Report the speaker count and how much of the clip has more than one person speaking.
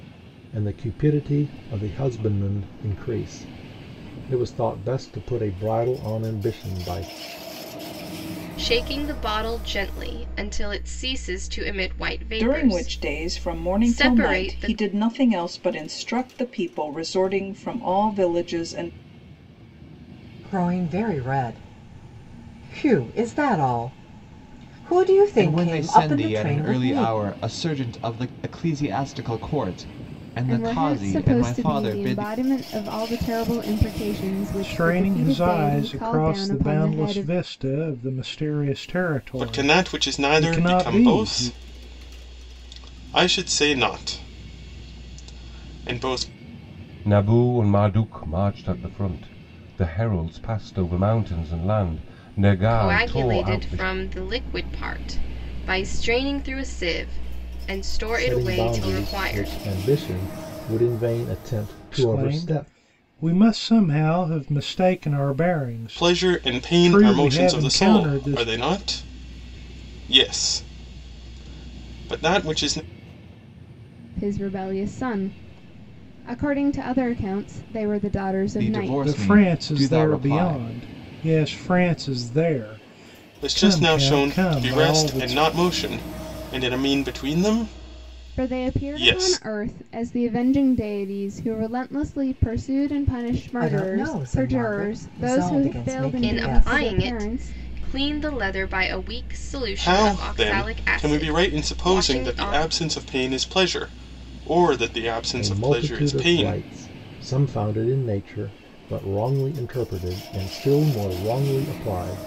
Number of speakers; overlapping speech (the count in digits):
9, about 27%